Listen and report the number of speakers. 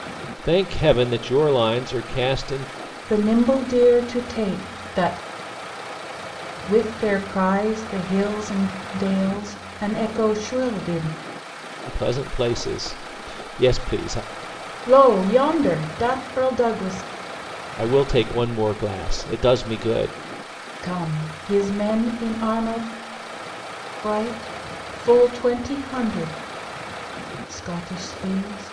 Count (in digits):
2